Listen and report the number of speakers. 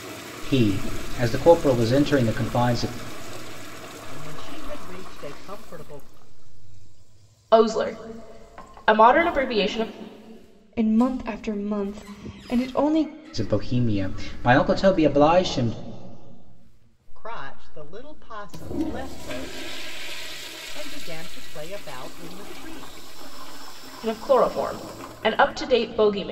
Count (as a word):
four